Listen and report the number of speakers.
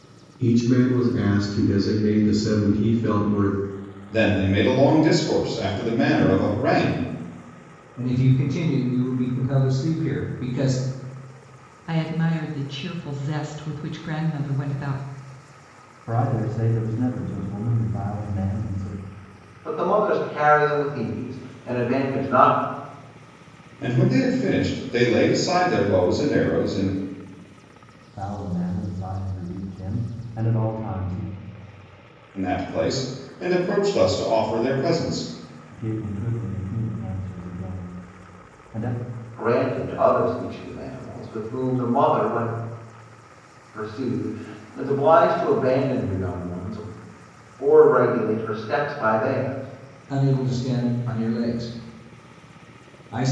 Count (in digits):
6